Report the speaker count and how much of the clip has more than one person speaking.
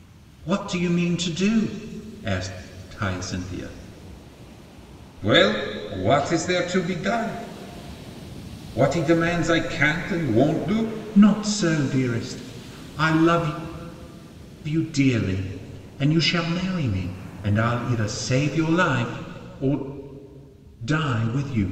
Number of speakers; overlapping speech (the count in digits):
1, no overlap